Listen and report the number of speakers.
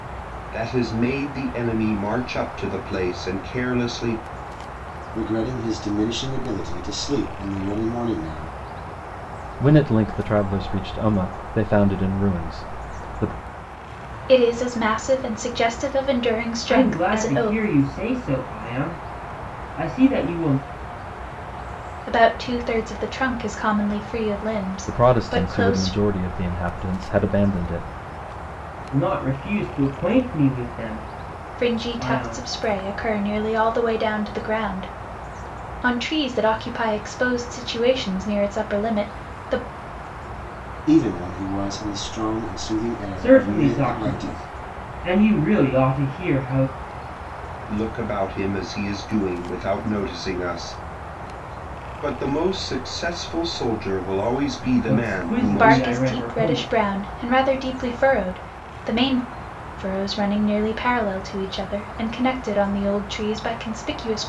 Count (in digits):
5